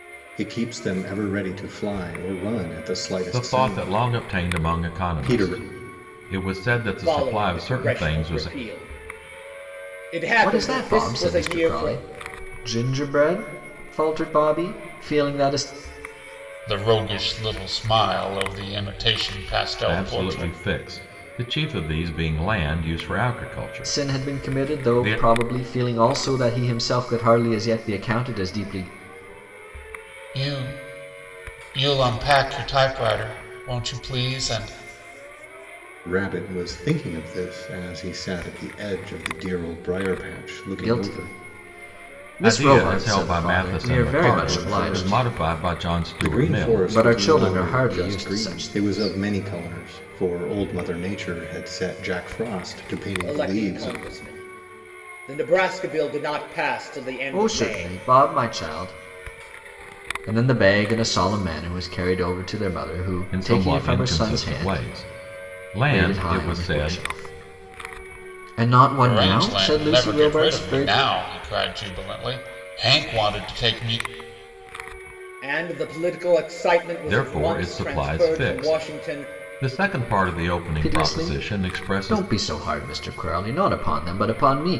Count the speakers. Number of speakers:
five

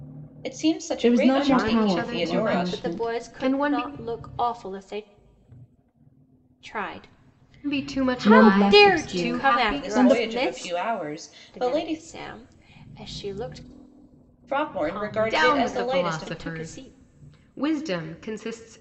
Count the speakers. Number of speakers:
four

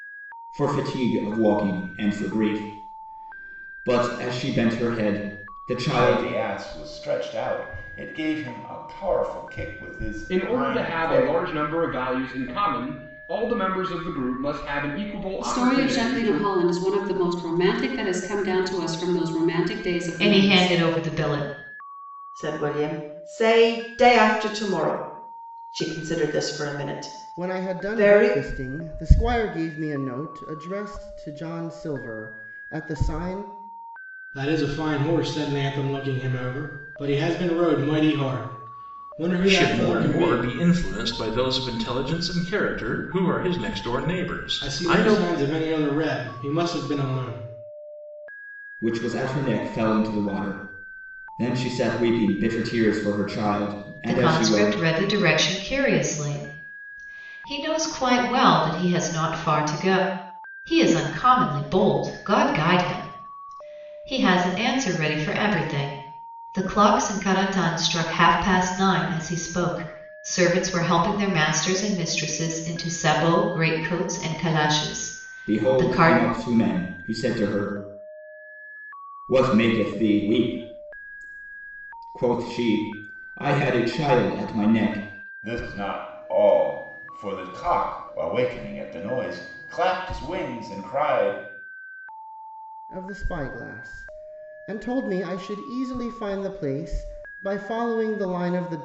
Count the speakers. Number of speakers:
nine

